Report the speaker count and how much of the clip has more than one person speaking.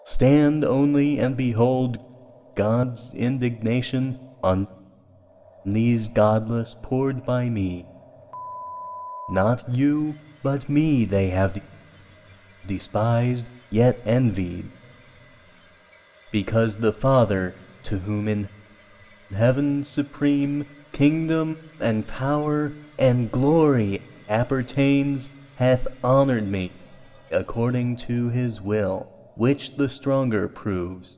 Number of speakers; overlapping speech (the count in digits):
1, no overlap